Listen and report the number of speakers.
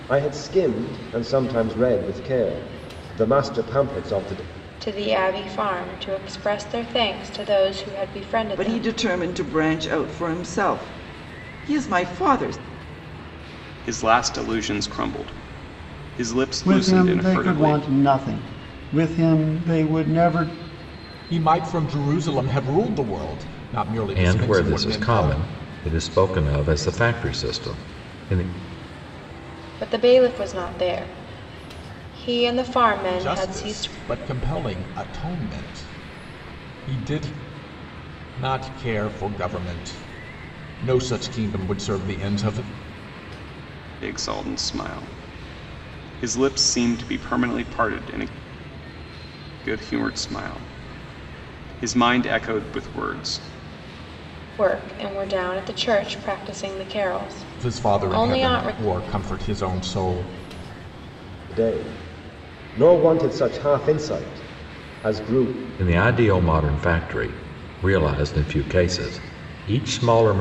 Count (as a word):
seven